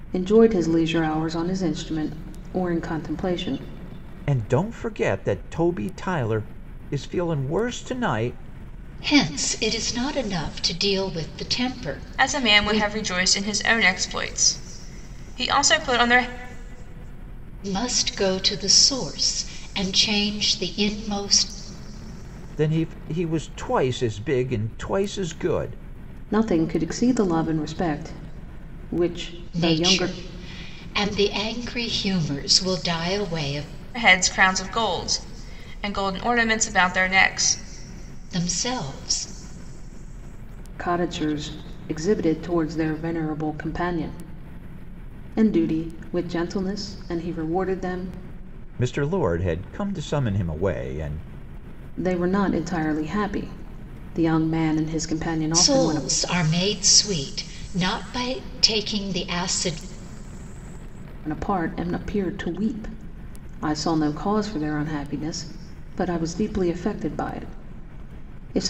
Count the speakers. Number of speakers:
4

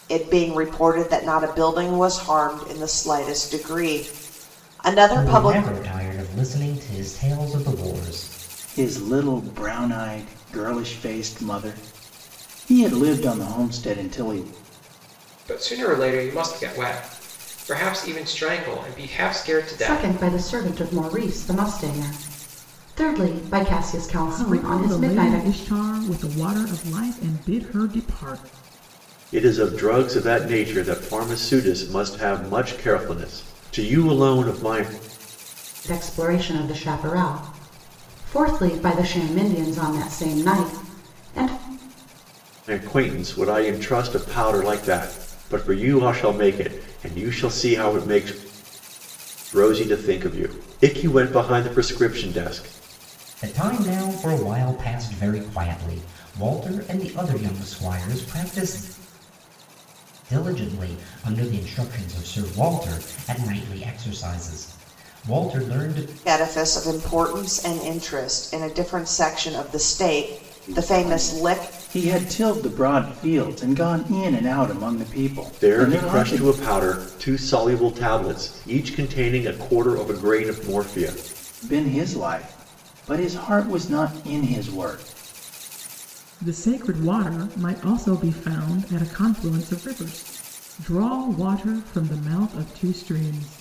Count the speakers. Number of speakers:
7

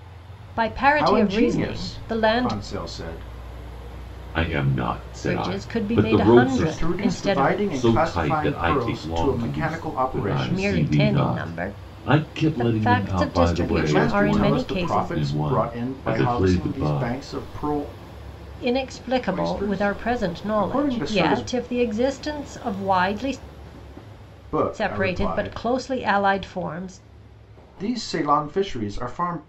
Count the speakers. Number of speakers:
3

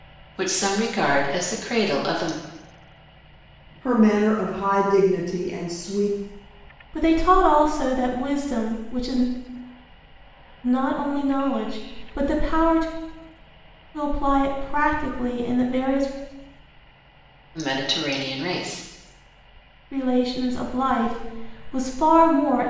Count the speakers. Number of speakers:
3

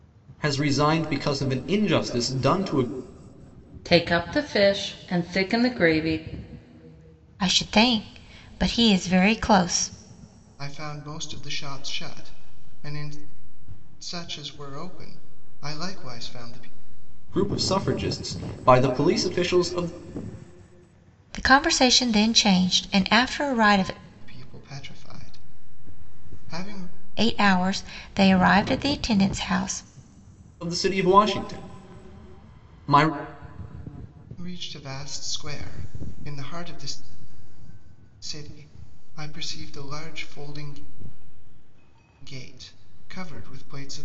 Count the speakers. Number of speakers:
4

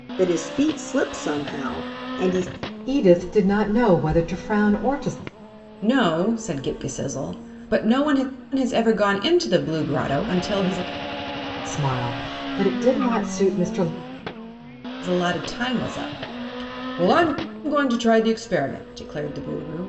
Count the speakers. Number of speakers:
3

